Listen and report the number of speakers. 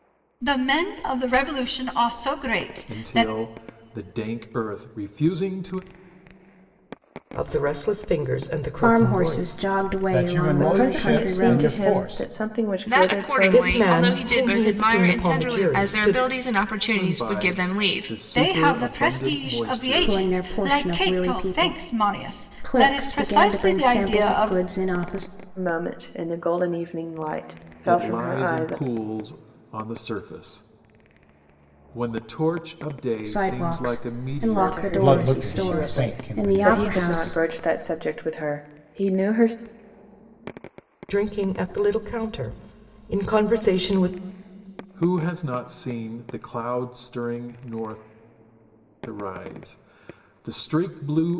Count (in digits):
7